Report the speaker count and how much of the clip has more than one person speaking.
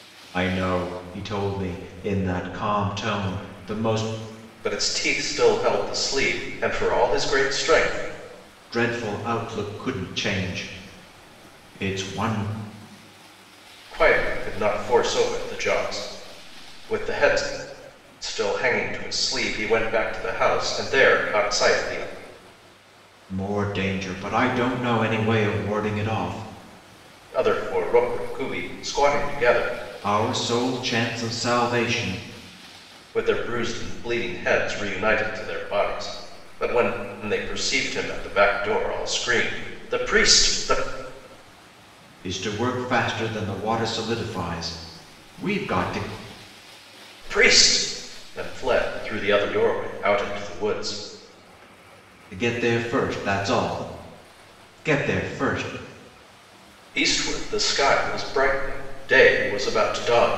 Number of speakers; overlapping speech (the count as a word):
two, no overlap